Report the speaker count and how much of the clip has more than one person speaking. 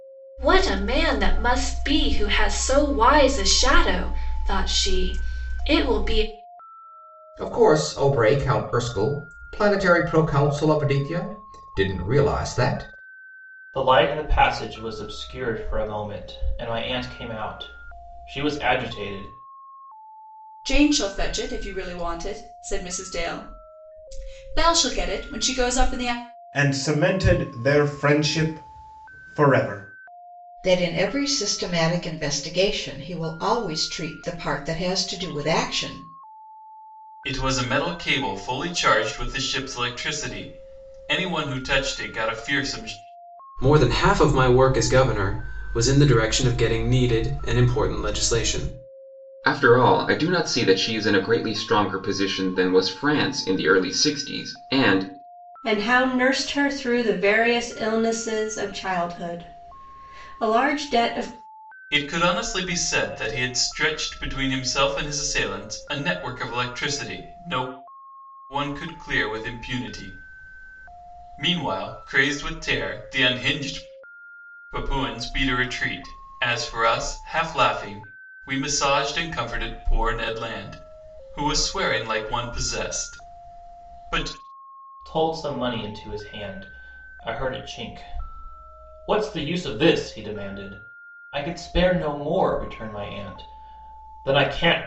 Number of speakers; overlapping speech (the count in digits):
10, no overlap